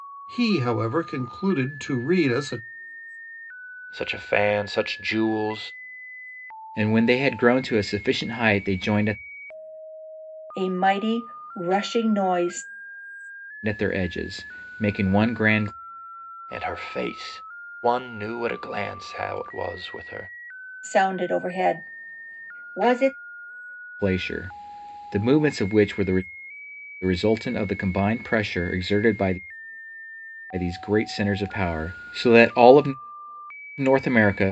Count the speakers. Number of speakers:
4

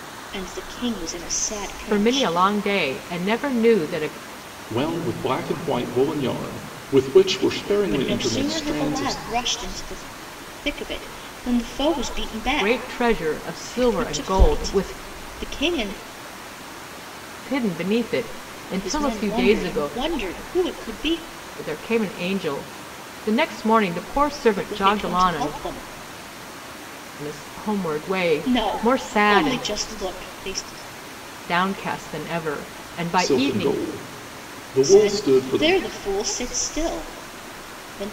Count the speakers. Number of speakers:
3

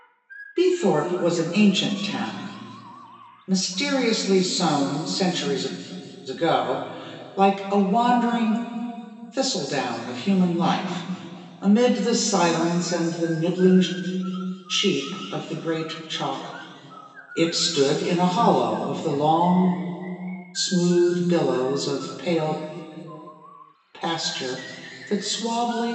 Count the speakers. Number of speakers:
1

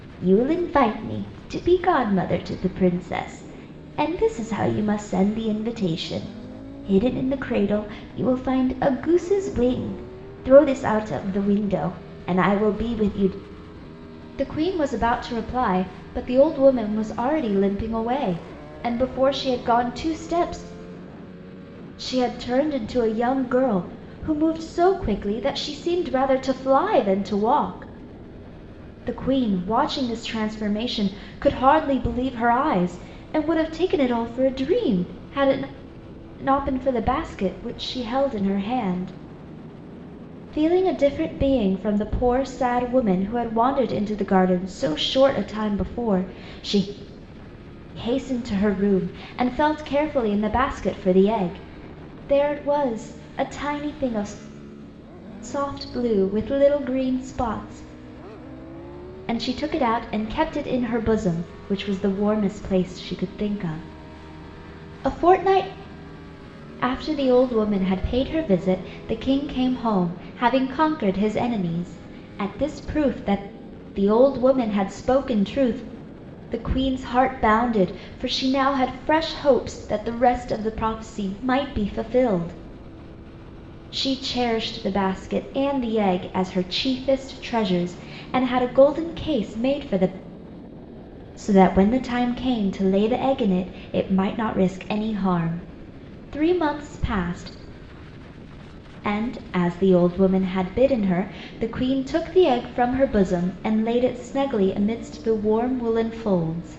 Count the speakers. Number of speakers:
1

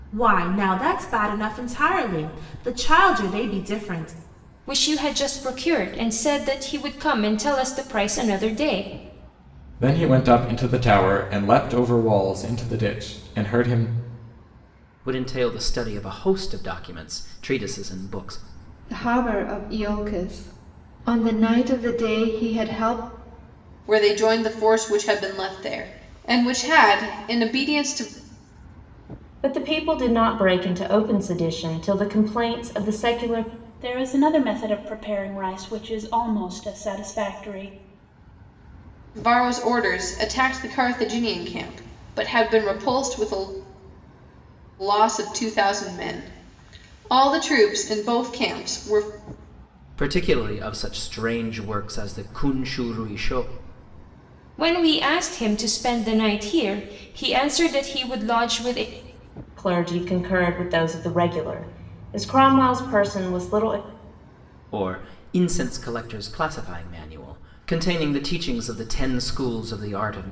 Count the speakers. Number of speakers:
8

